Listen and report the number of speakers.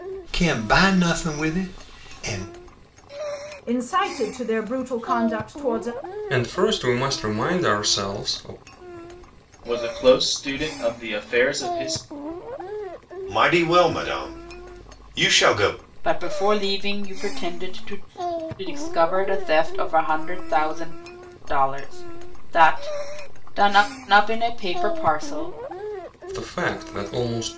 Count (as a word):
six